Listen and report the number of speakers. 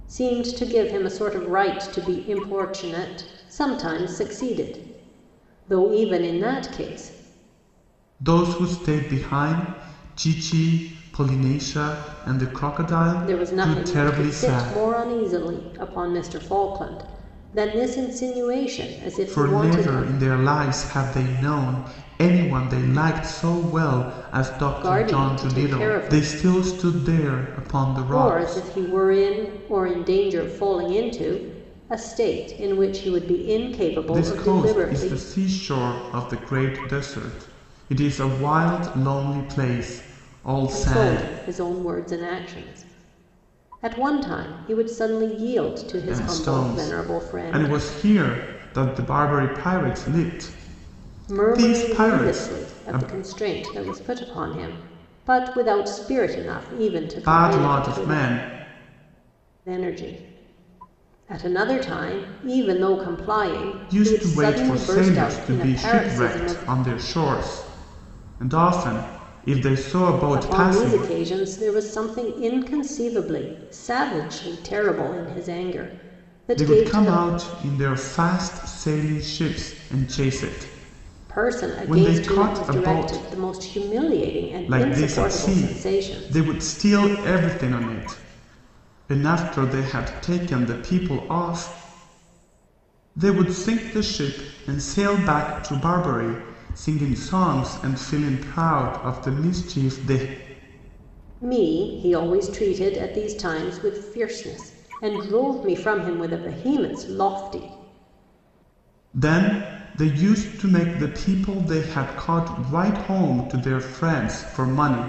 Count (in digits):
2